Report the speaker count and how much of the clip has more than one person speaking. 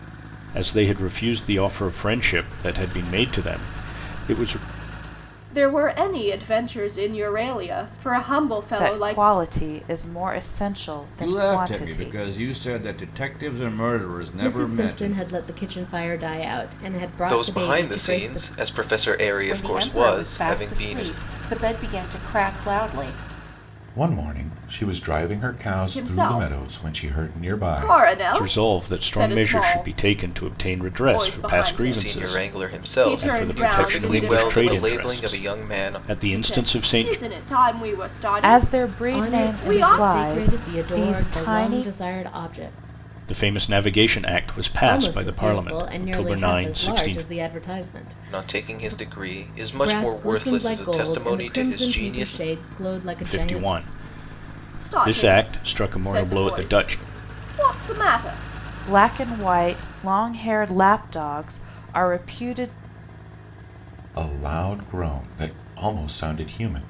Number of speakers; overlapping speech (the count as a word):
eight, about 40%